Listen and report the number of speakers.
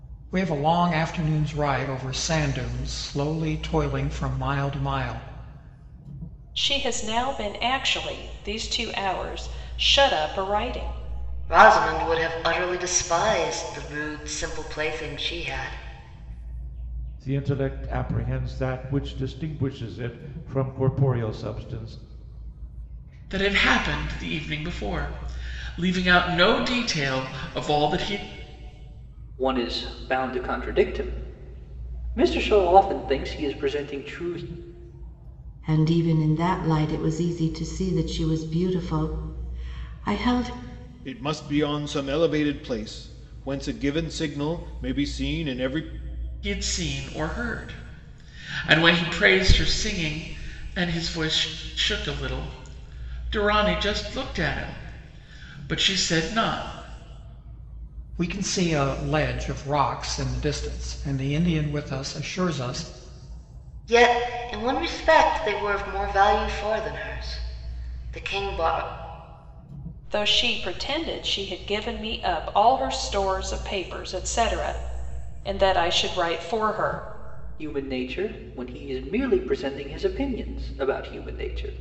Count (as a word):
eight